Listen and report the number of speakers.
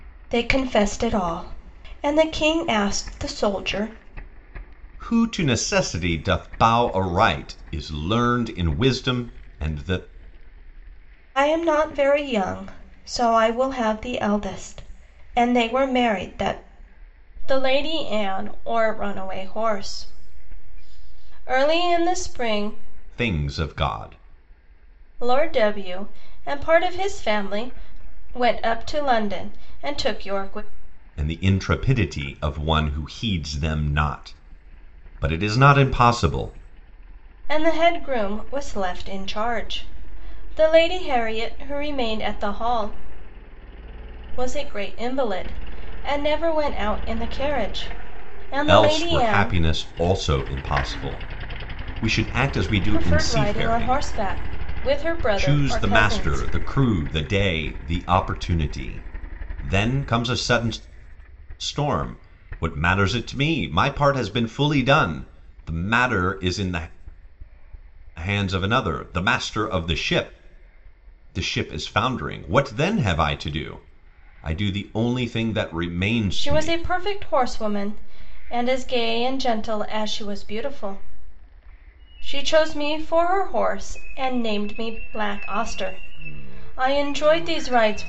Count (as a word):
two